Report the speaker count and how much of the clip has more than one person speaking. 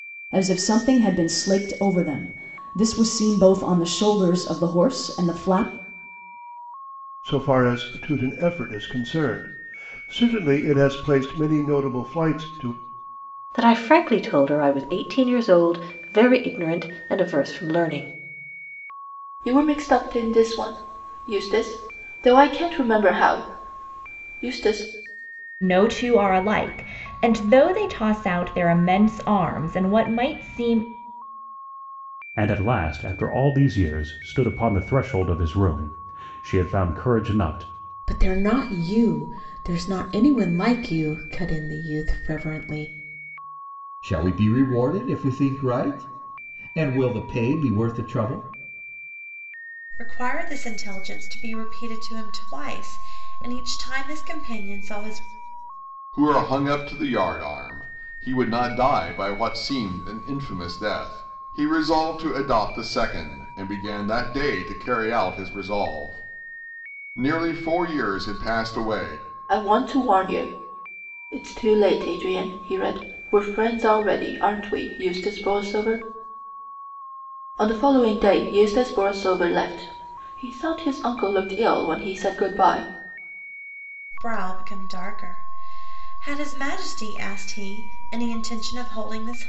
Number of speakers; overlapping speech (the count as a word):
ten, no overlap